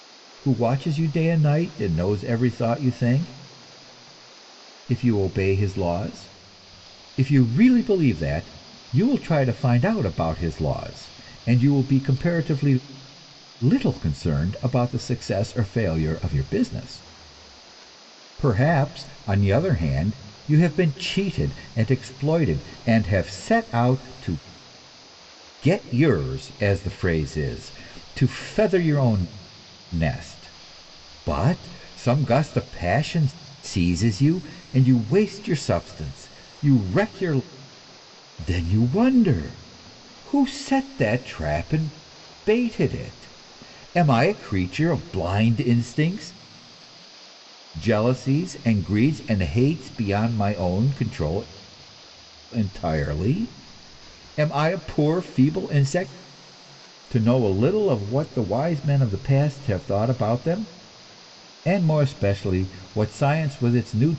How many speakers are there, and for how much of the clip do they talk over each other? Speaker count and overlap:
1, no overlap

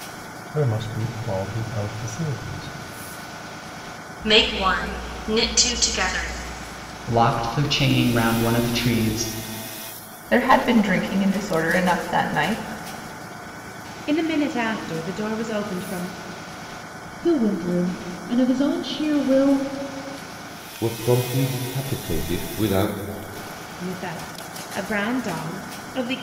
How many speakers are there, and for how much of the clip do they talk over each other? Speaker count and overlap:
7, no overlap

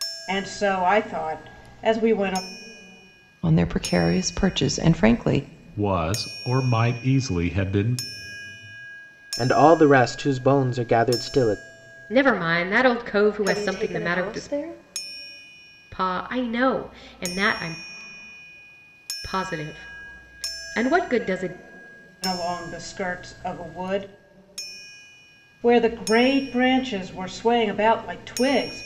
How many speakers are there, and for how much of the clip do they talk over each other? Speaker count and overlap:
6, about 4%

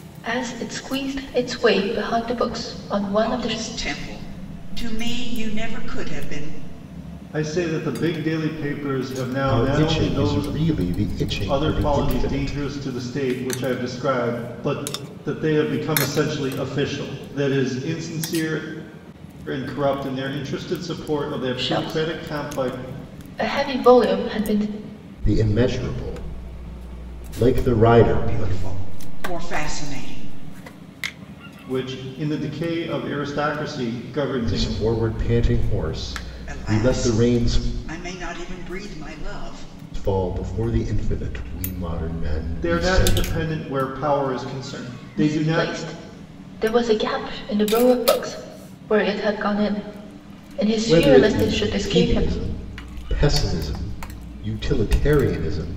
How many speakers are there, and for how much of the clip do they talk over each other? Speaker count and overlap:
4, about 16%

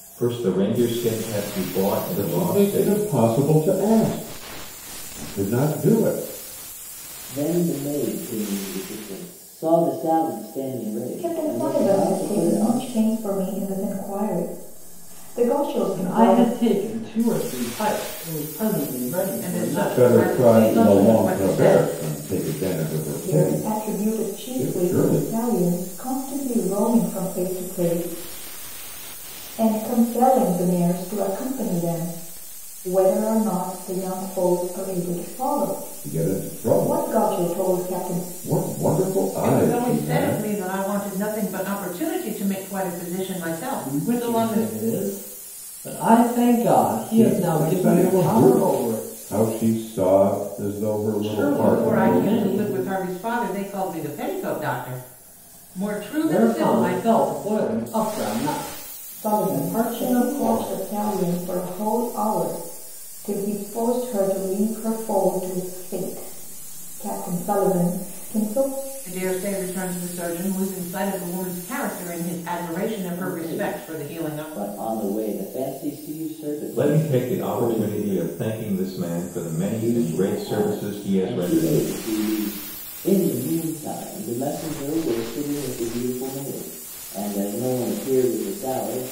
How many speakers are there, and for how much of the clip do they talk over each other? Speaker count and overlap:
6, about 26%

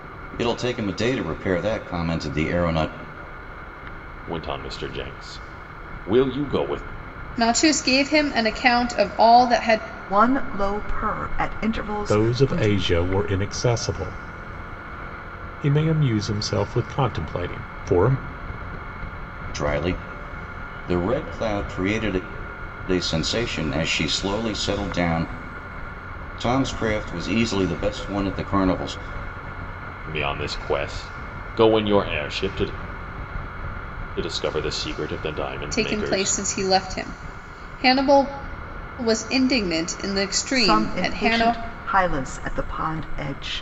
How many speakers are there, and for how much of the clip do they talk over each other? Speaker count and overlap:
5, about 5%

